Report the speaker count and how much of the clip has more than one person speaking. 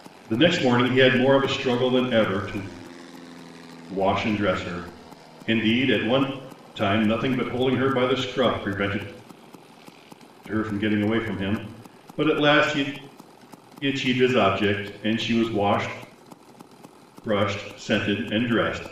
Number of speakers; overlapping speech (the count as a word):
one, no overlap